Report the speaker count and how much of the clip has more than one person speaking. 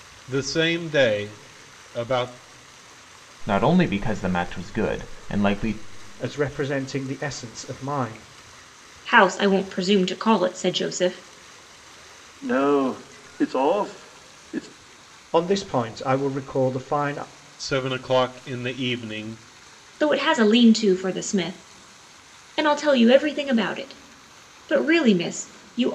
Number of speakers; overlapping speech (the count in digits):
5, no overlap